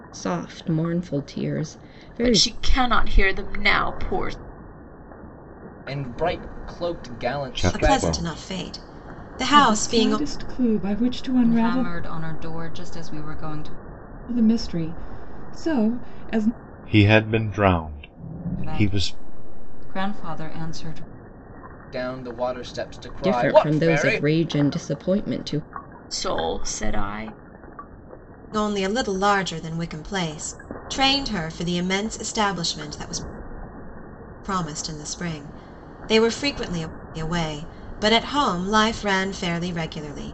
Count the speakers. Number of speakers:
7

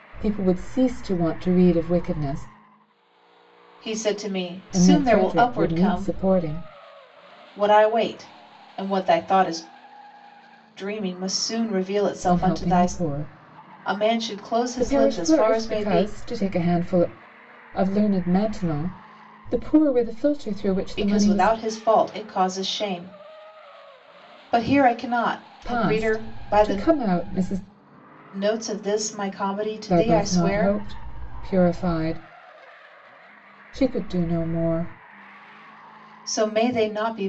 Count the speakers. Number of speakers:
2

